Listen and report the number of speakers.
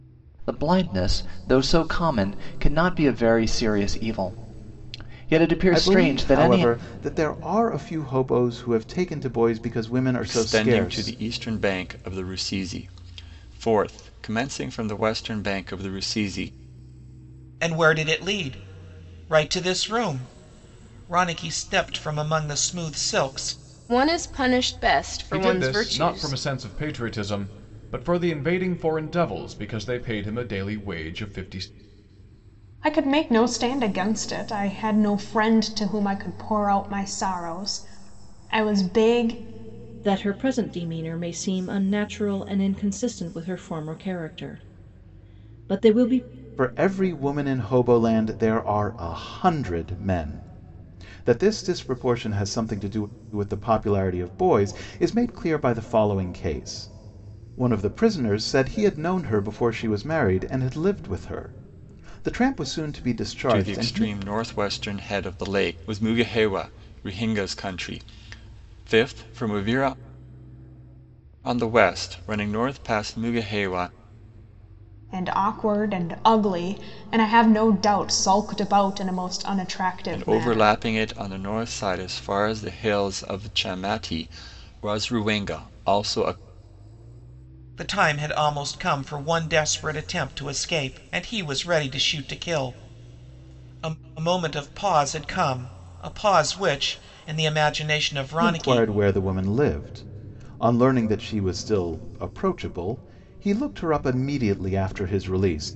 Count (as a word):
eight